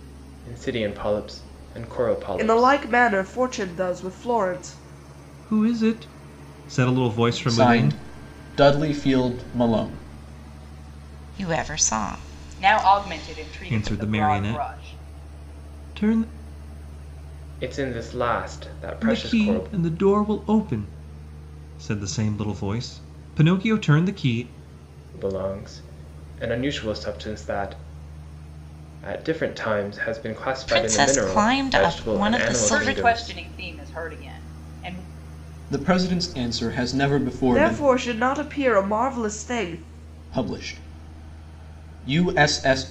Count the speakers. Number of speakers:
6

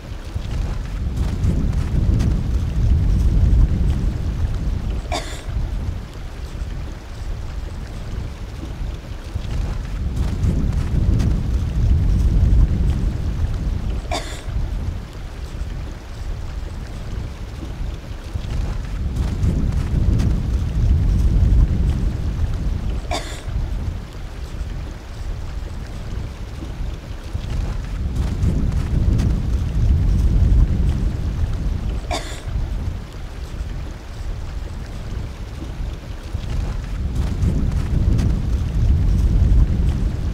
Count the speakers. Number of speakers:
0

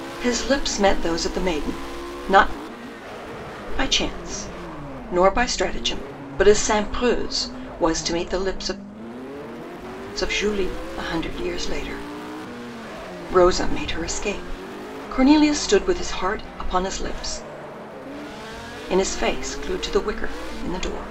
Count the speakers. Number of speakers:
1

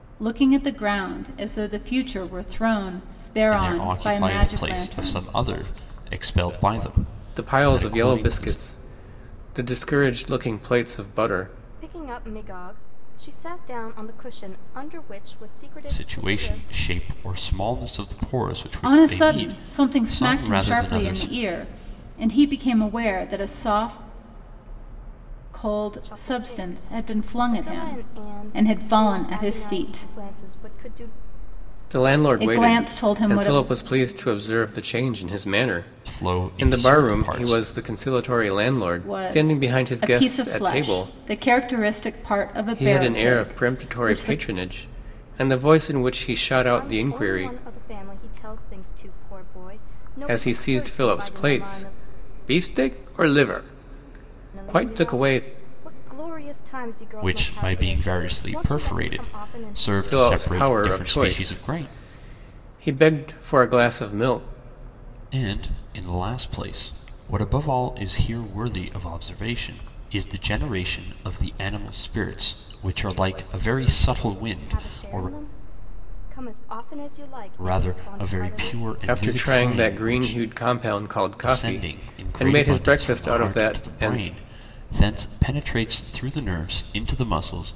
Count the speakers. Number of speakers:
4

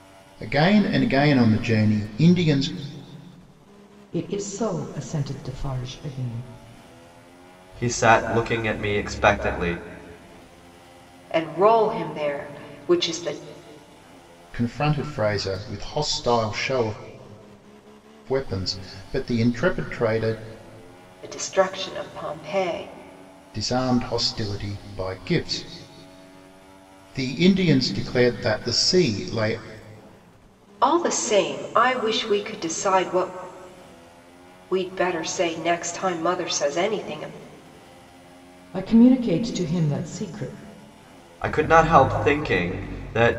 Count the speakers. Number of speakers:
4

